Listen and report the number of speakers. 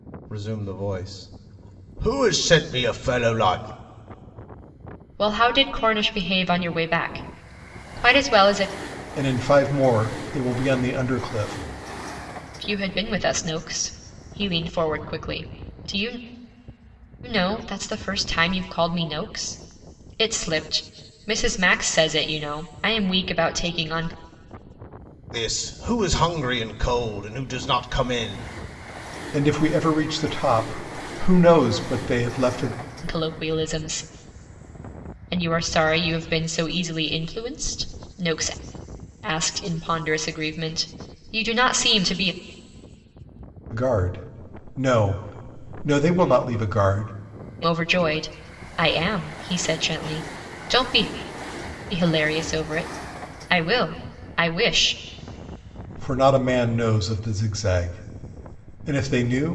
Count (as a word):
three